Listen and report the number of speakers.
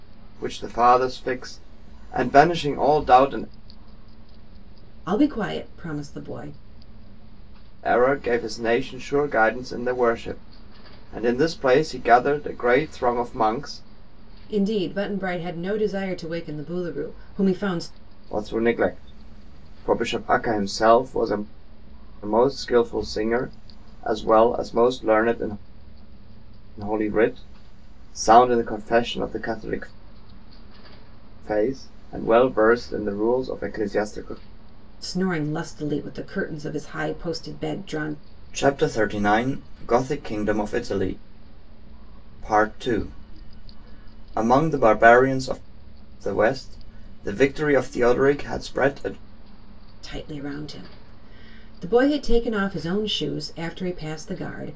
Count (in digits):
2